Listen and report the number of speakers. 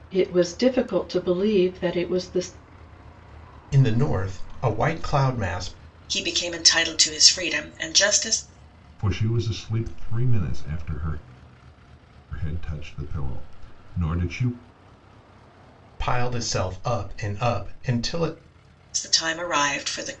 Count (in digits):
4